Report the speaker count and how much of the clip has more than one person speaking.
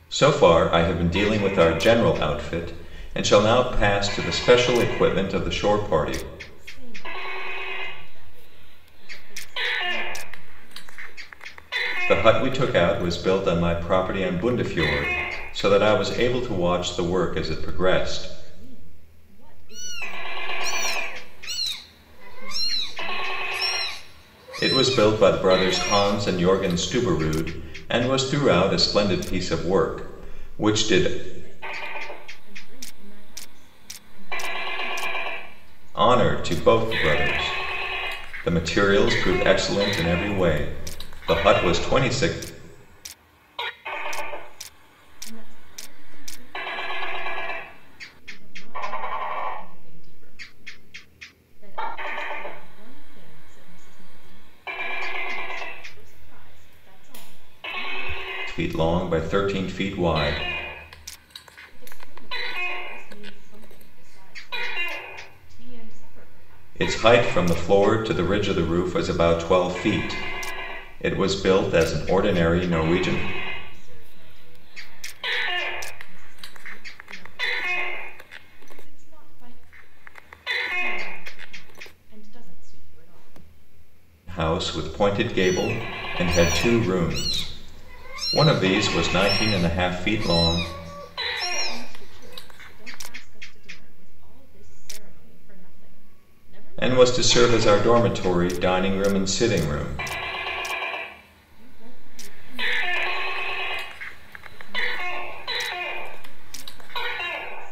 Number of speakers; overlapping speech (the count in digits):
2, about 6%